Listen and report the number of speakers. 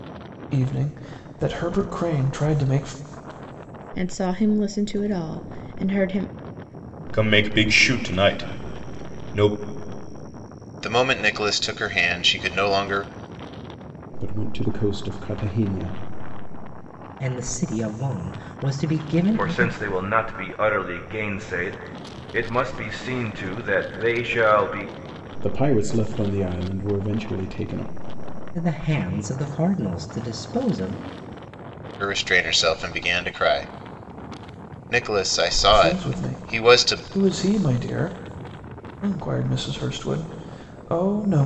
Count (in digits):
7